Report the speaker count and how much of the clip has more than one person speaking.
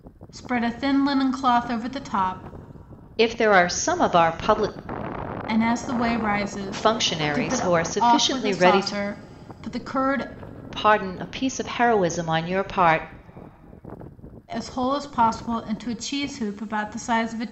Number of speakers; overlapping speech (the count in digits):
2, about 12%